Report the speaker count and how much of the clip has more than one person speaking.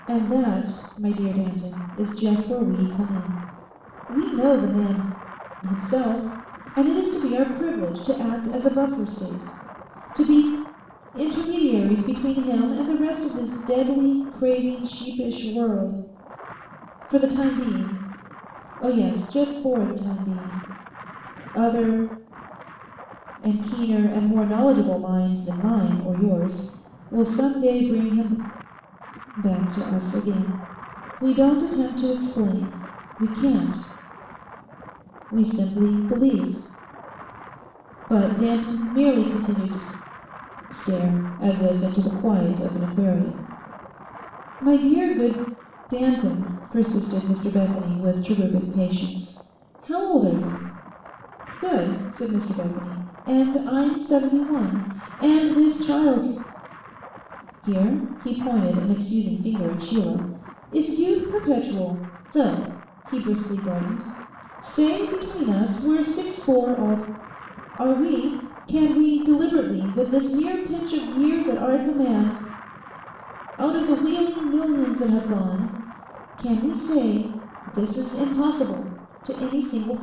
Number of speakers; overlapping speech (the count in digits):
1, no overlap